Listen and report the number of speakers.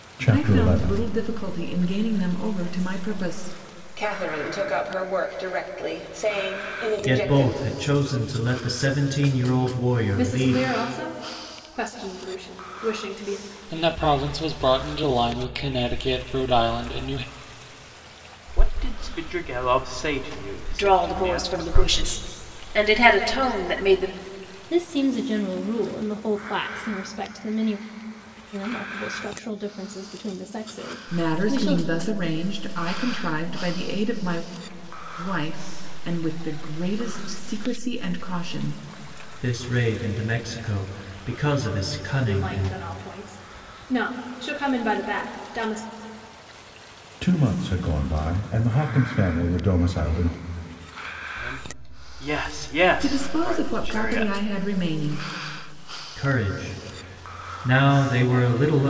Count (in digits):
9